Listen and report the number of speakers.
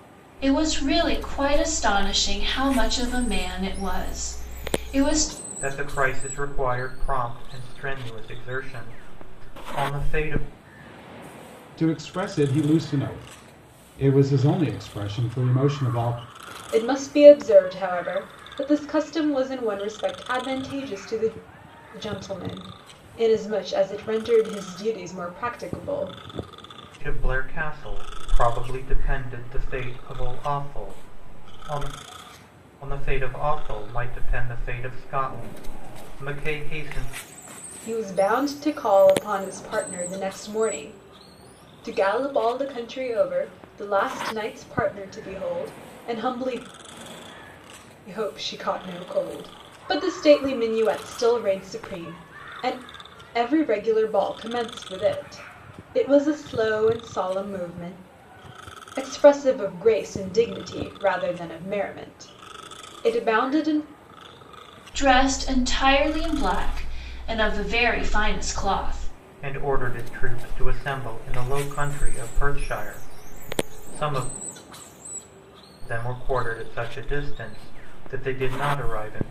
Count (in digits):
4